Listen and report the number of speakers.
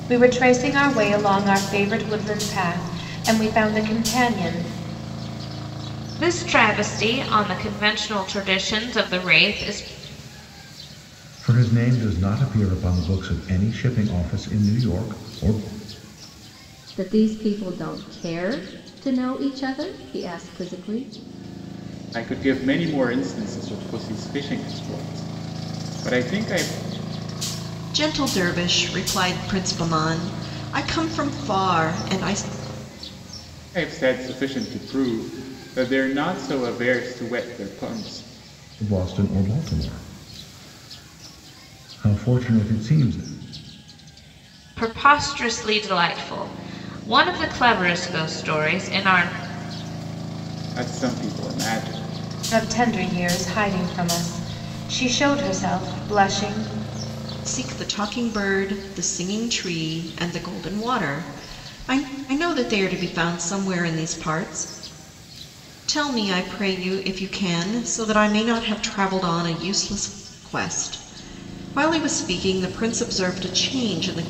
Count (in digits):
6